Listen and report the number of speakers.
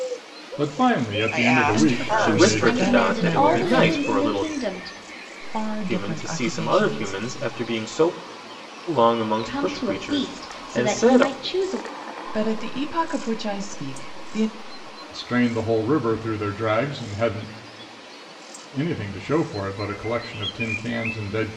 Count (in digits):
5